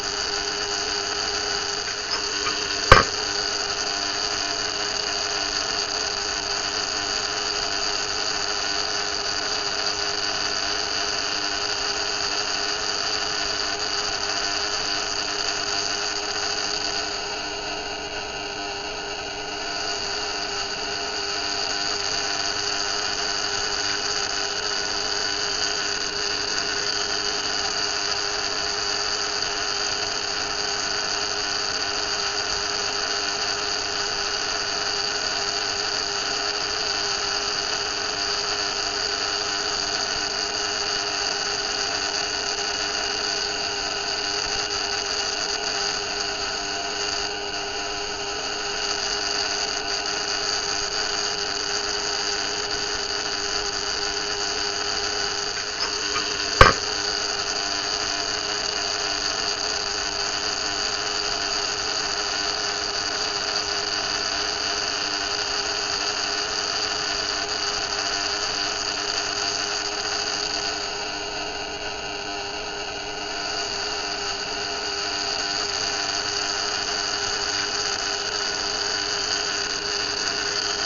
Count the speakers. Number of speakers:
0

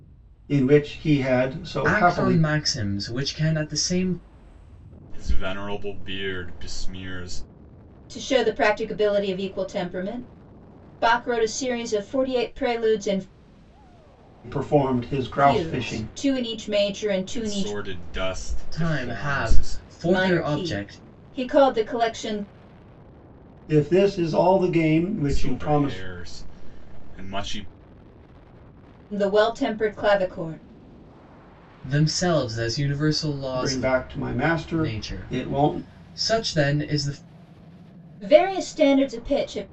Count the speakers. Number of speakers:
4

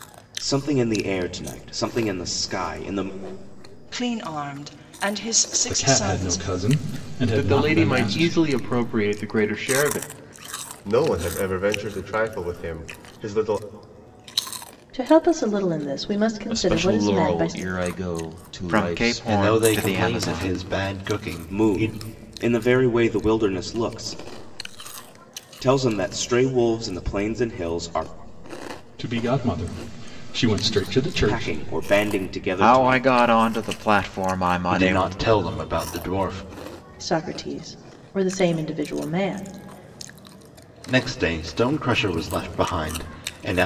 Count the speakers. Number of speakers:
9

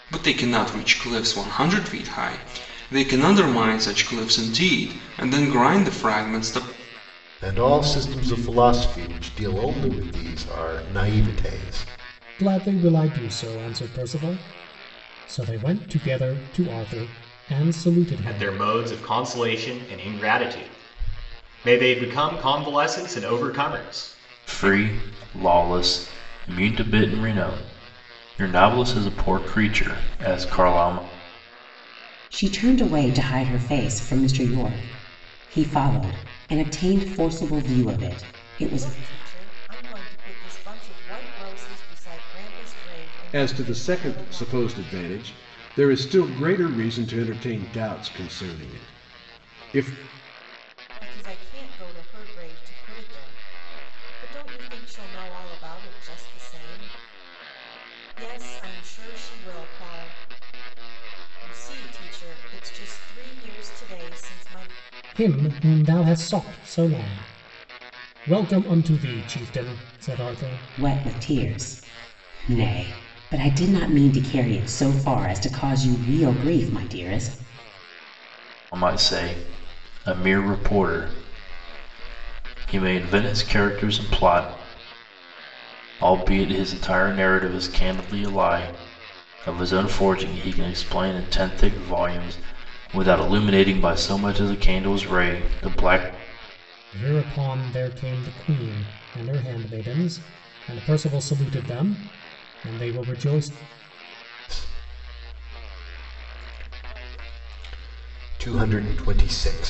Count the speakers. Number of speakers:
8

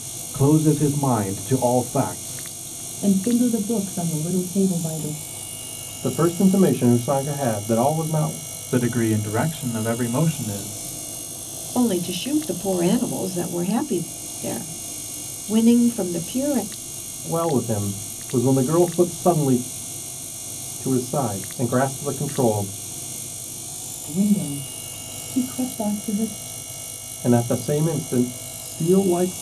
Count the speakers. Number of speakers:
5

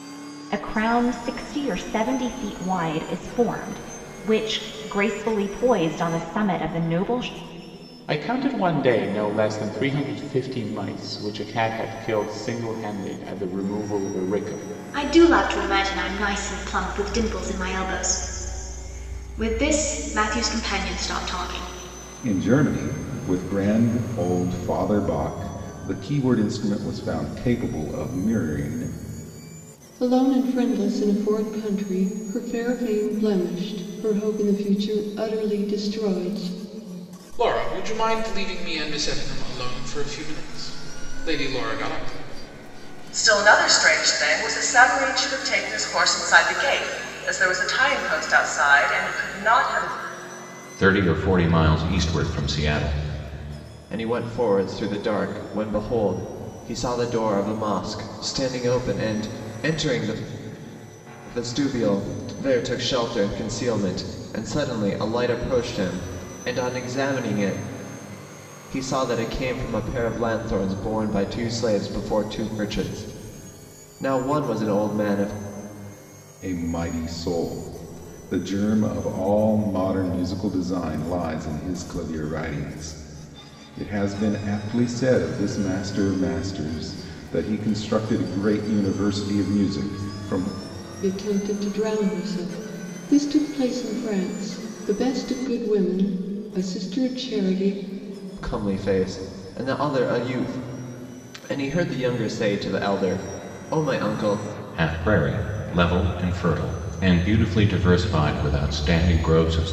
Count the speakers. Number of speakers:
9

